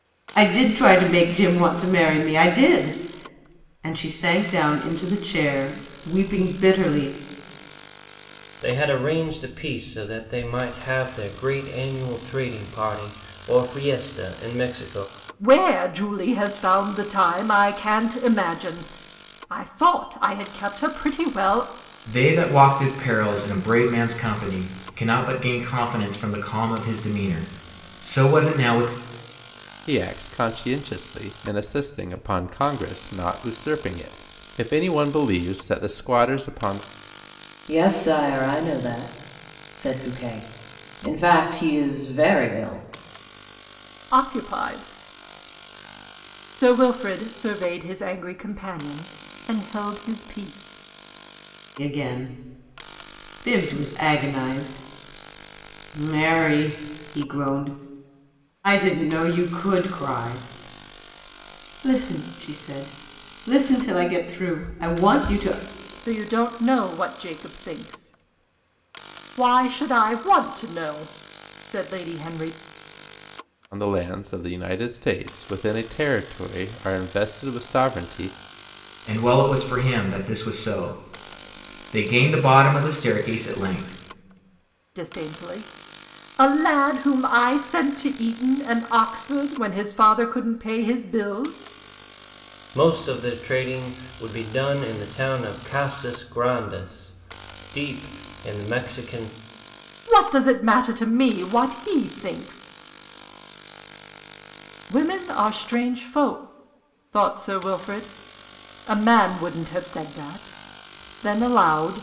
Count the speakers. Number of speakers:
6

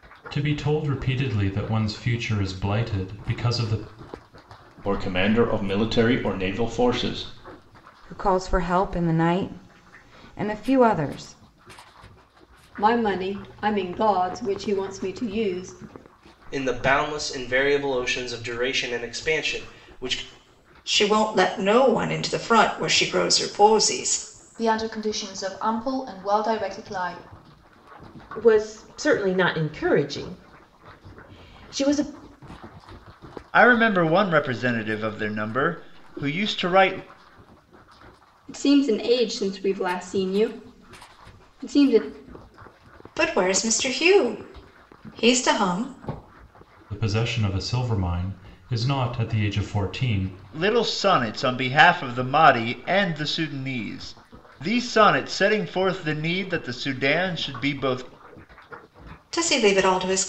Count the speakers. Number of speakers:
10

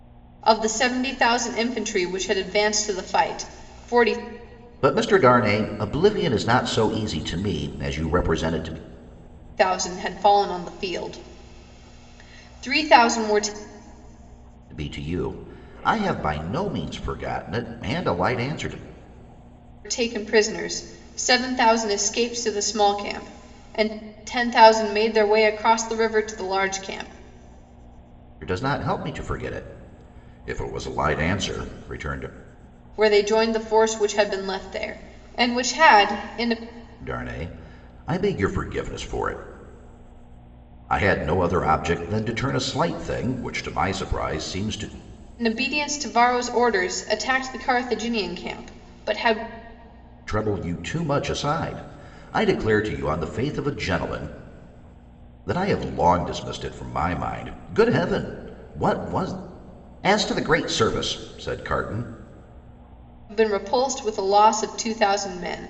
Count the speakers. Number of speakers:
2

